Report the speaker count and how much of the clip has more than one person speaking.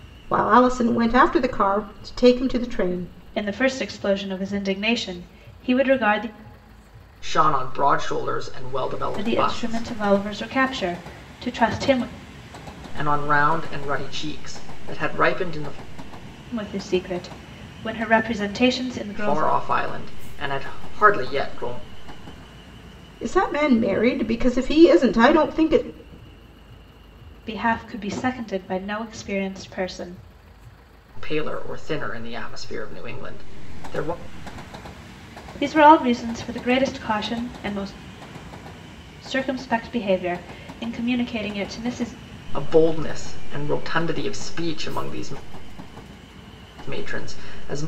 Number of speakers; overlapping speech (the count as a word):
three, about 2%